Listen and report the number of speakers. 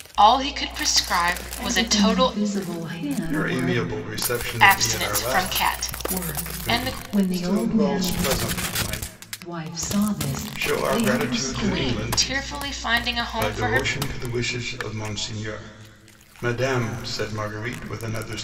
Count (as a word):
three